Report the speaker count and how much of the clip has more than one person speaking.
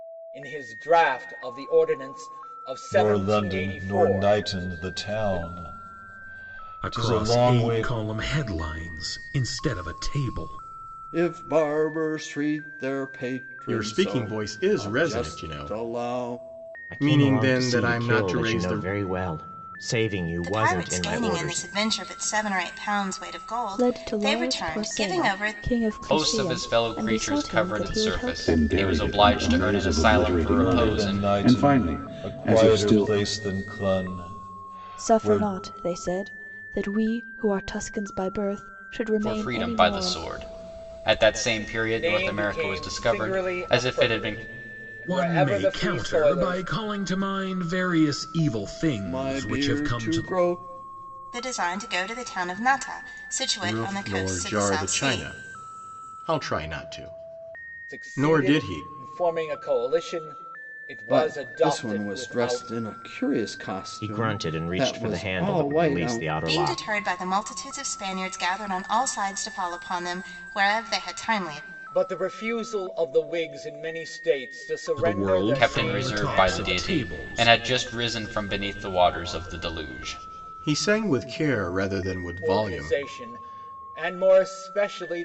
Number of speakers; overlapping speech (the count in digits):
10, about 42%